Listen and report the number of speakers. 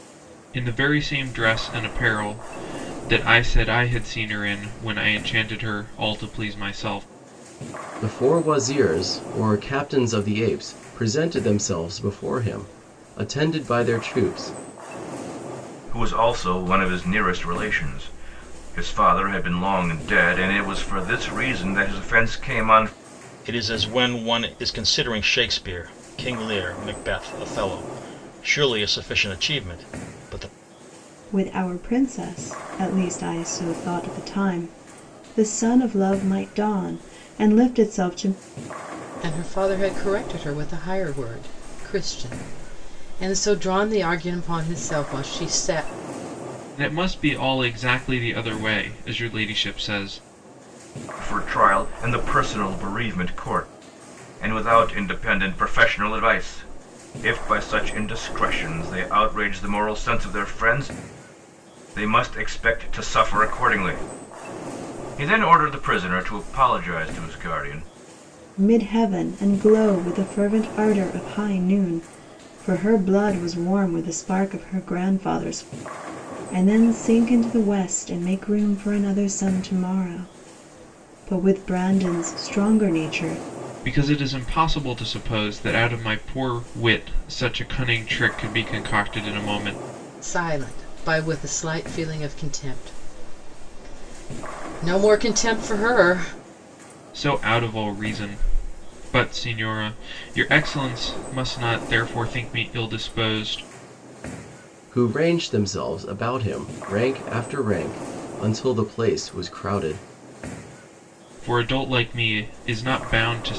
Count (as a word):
six